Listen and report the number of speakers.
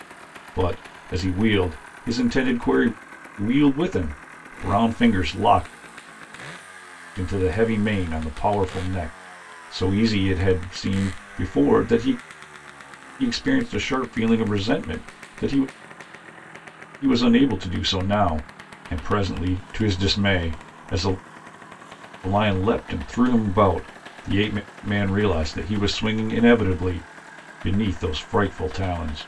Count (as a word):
one